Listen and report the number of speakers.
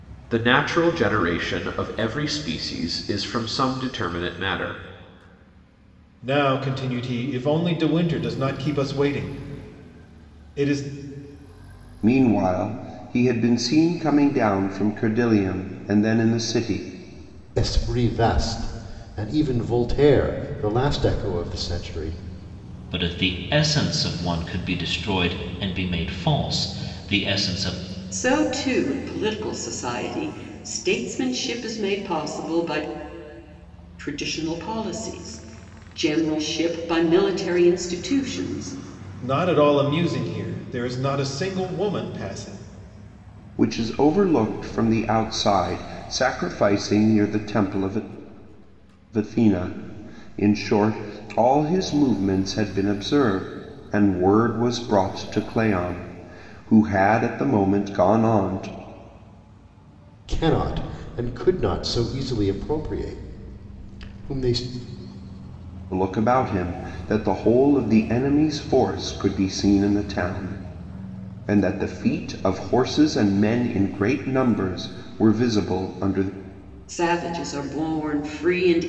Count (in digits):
6